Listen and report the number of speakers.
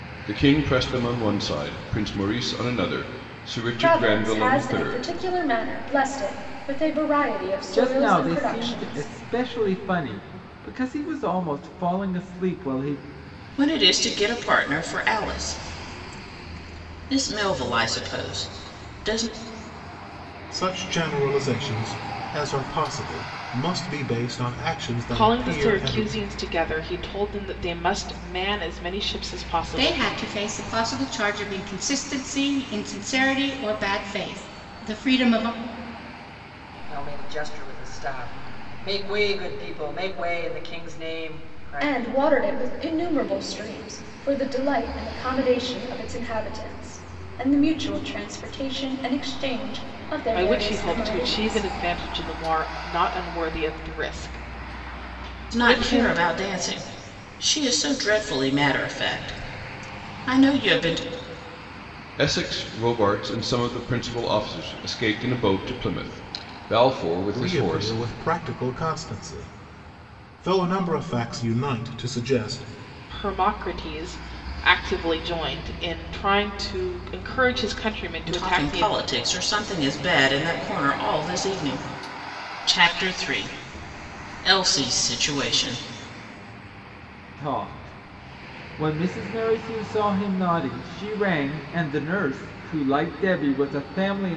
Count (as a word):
eight